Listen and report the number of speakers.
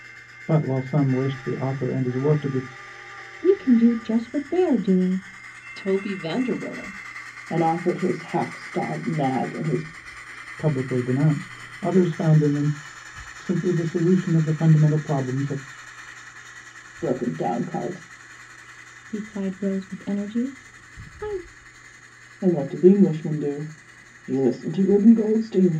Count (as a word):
four